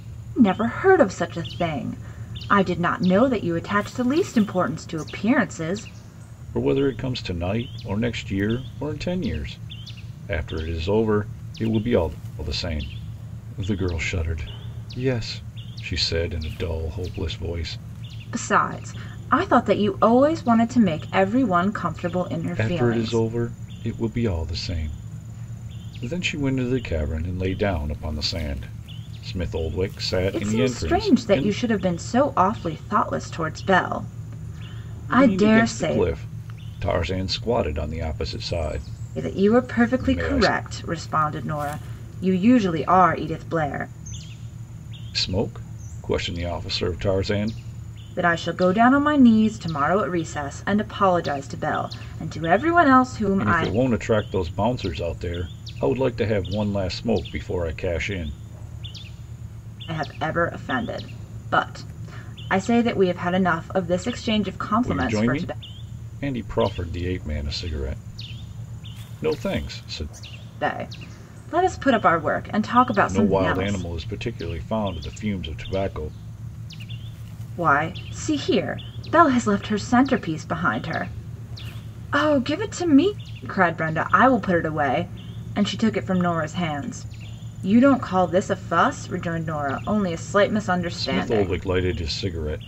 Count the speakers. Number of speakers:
two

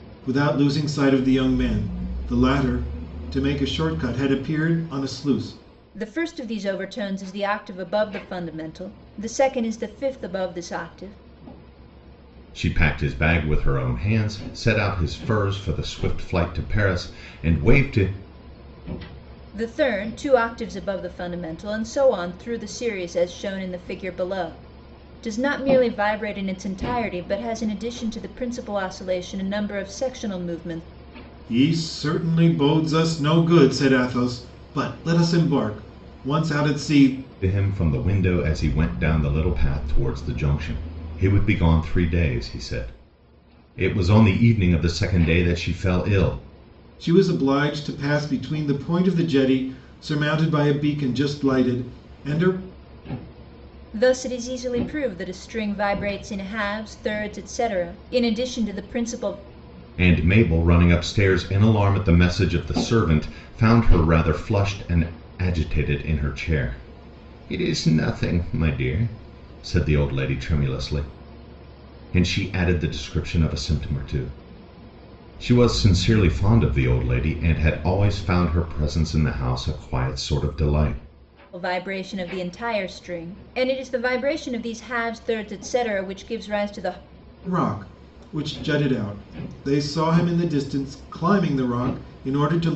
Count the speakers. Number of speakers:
three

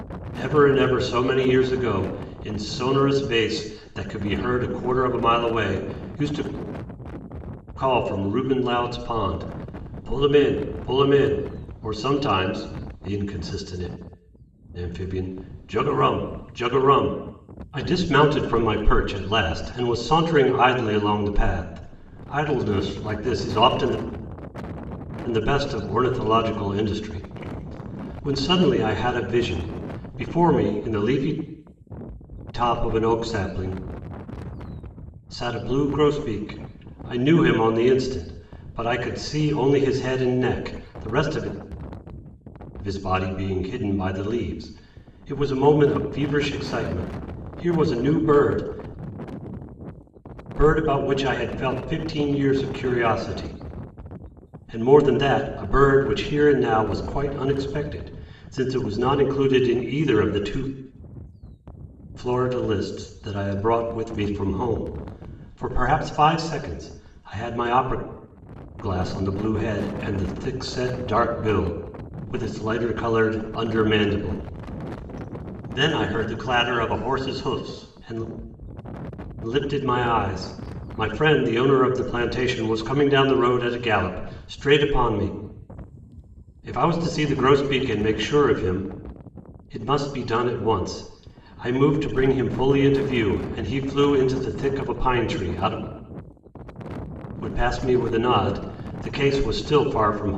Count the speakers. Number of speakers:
one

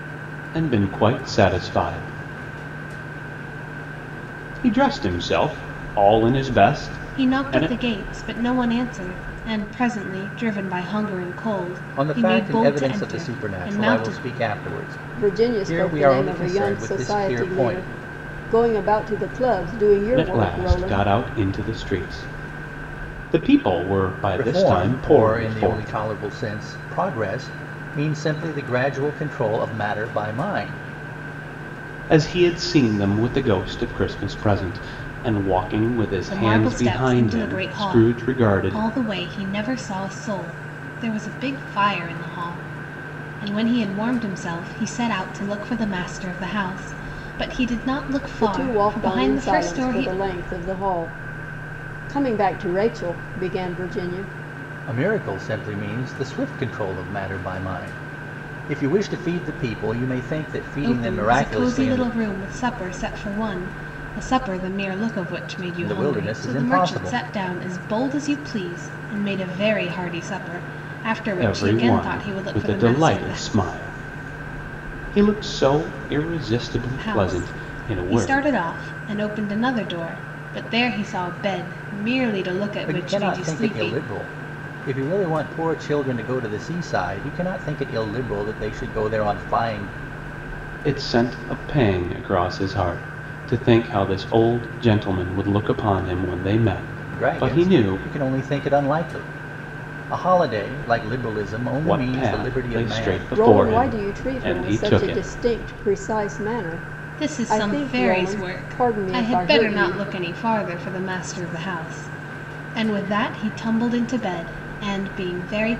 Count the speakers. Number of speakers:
four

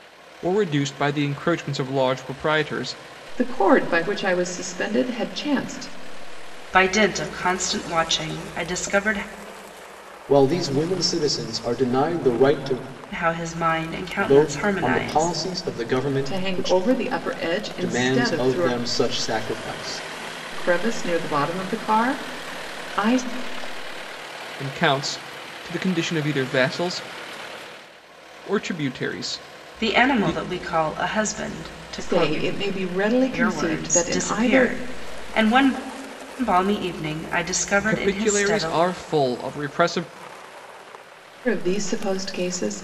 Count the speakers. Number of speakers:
four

